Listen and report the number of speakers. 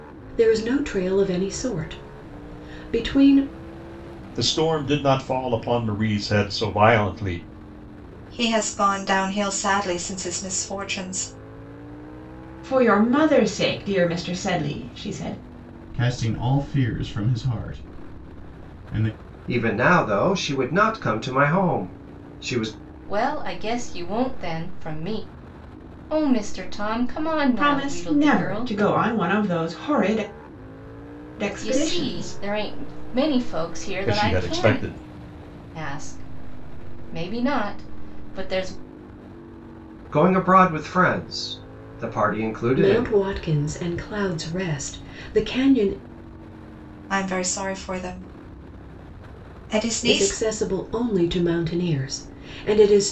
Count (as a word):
seven